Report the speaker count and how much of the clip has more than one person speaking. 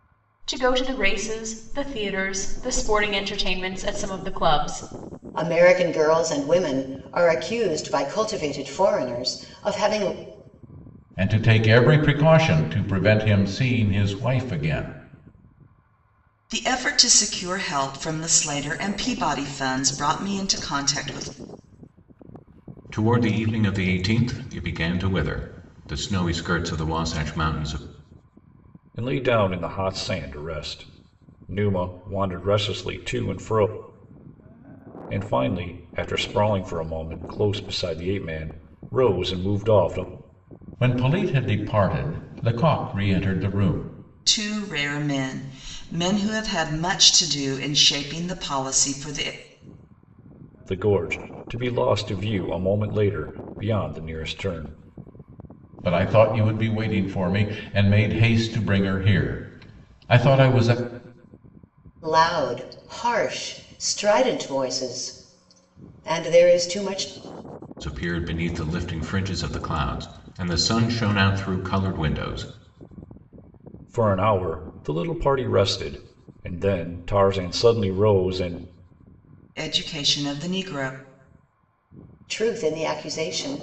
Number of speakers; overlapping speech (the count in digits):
6, no overlap